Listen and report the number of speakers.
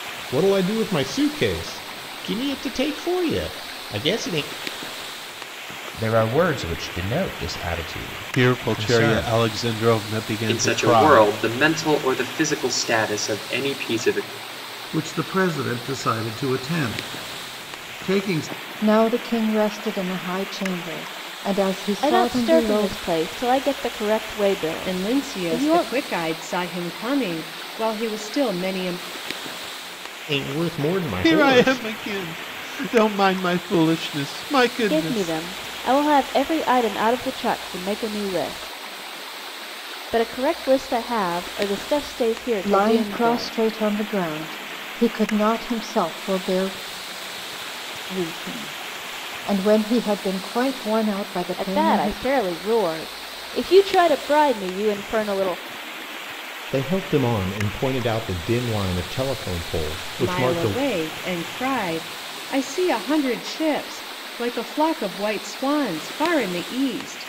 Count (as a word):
eight